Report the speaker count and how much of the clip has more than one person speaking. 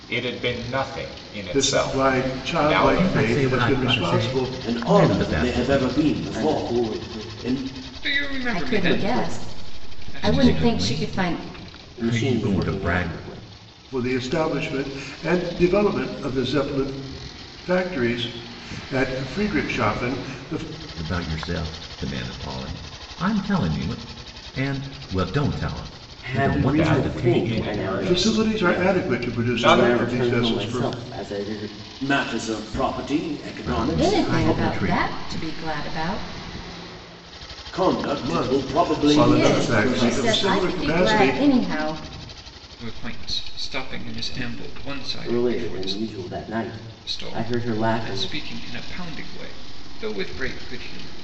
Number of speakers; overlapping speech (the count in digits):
7, about 43%